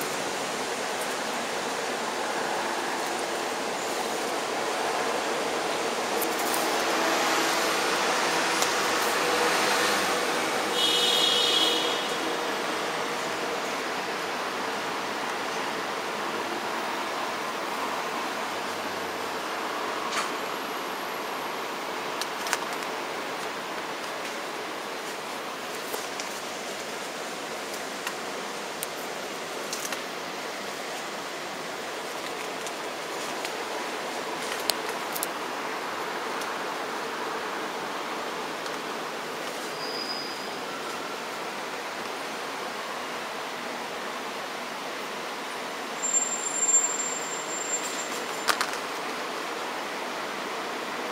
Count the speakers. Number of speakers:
0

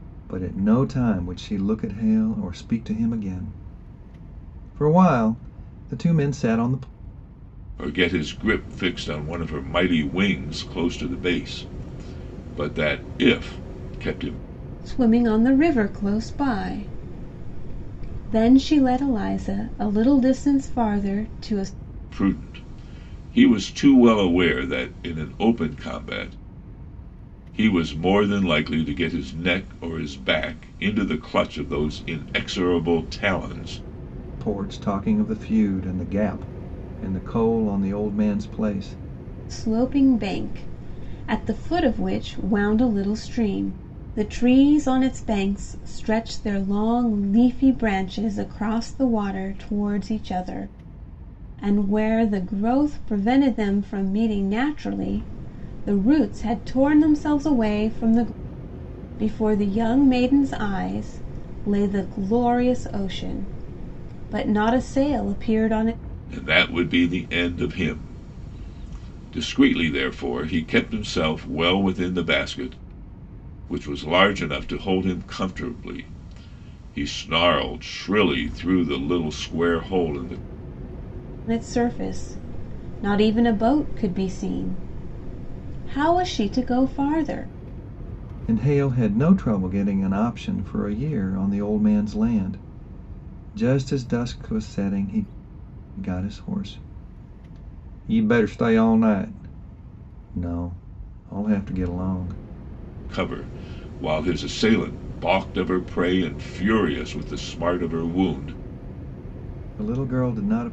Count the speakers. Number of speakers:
3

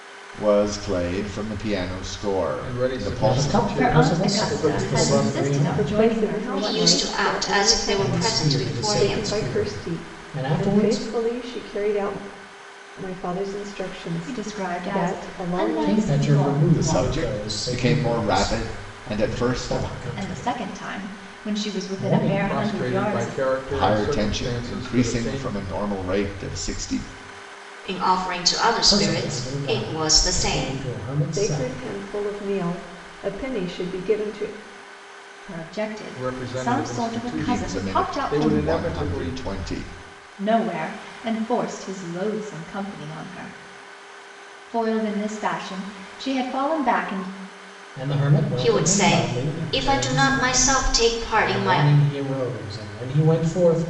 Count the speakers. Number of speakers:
6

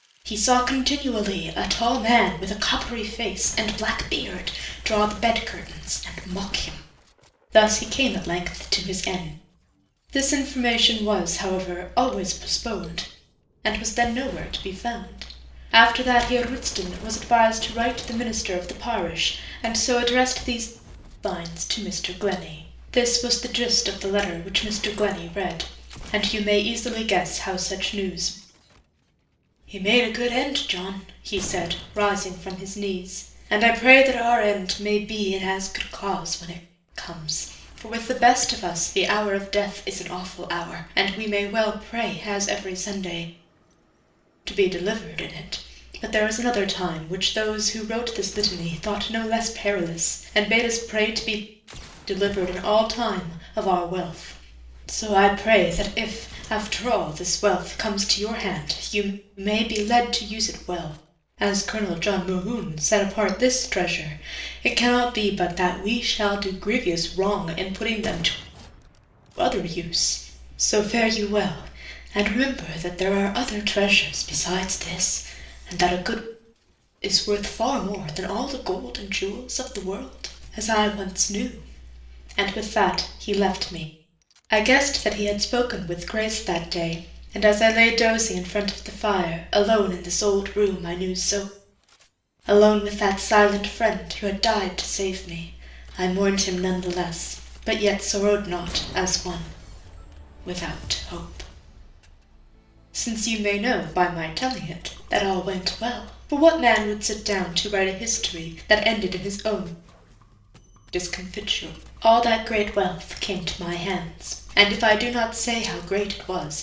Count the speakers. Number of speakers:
1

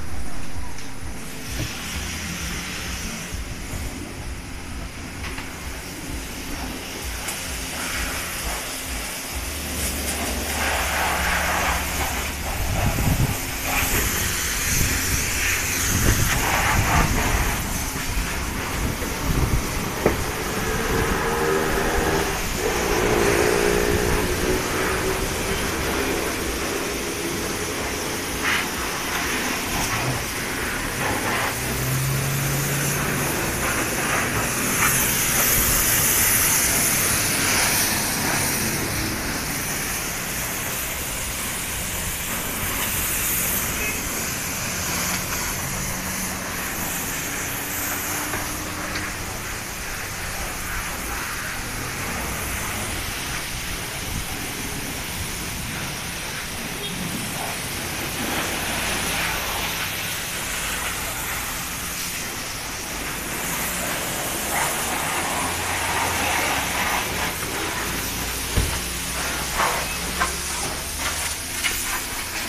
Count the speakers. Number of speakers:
0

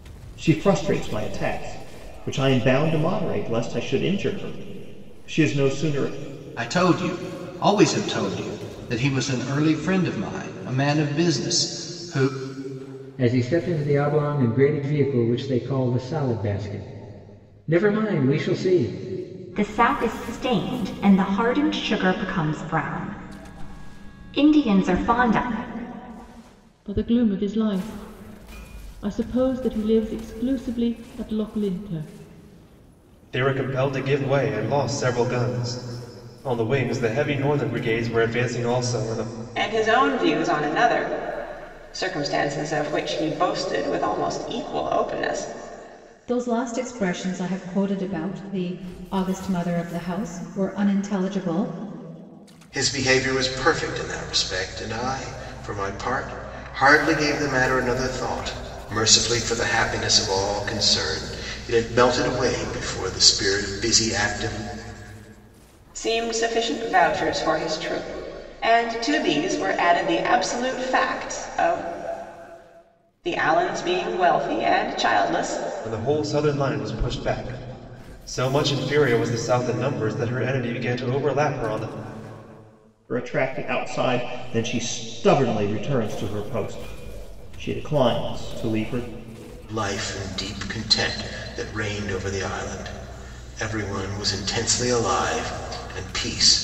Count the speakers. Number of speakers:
9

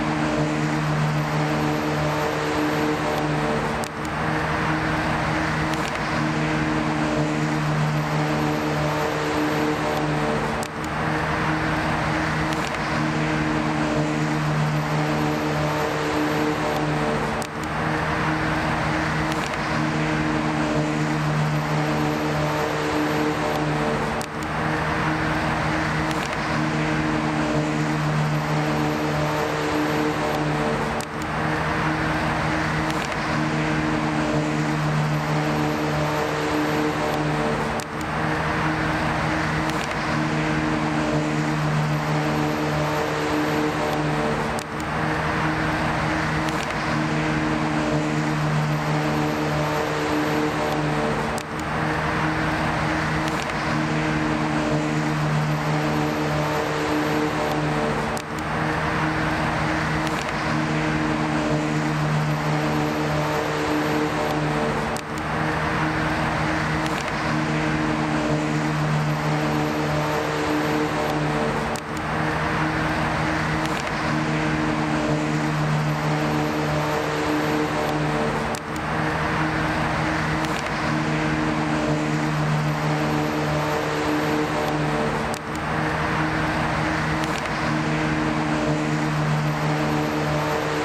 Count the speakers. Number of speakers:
0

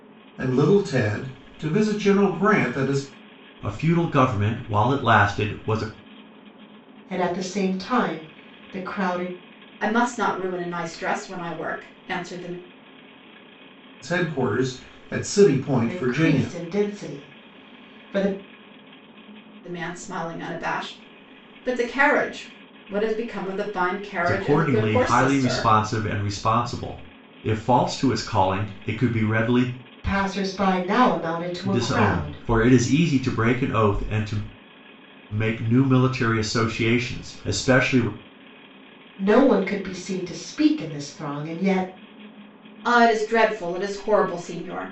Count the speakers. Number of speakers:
4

